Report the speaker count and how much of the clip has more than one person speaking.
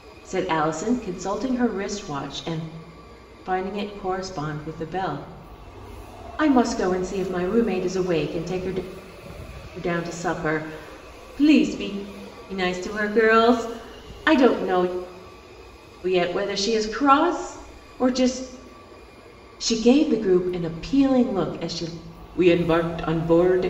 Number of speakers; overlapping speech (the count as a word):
one, no overlap